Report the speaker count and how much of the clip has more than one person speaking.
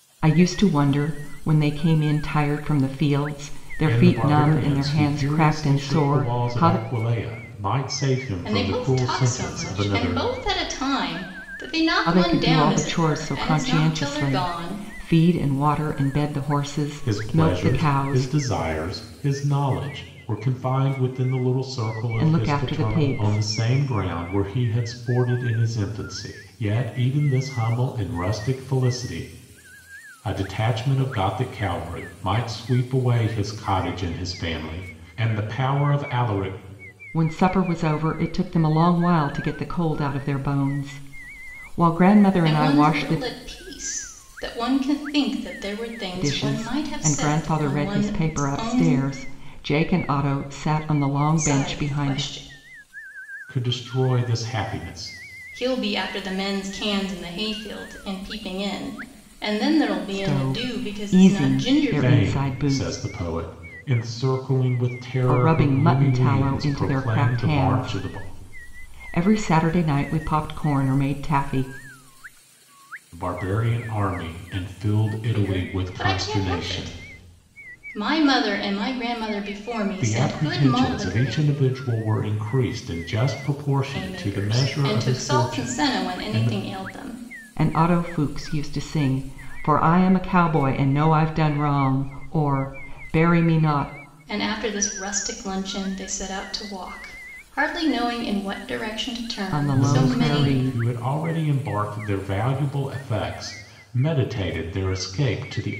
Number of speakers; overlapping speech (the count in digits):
3, about 26%